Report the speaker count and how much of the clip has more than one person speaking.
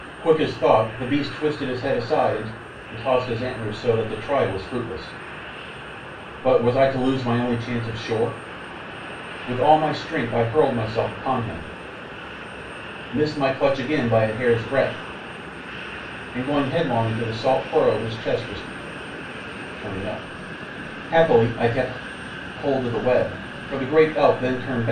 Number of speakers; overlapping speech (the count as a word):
one, no overlap